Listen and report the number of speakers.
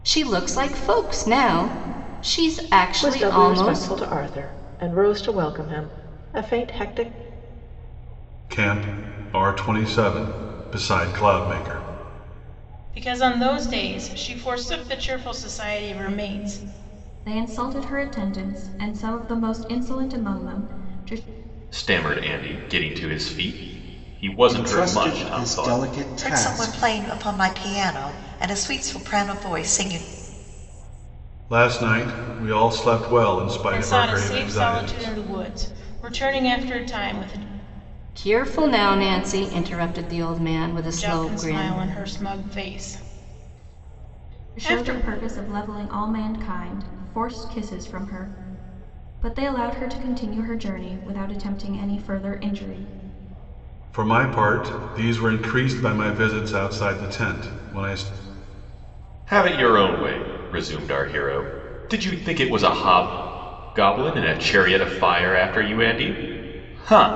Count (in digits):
8